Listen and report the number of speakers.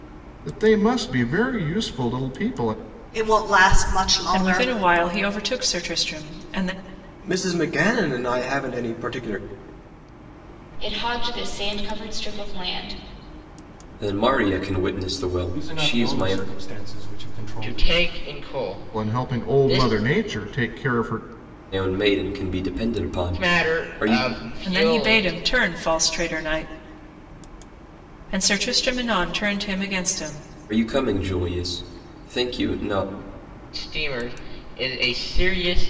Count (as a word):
eight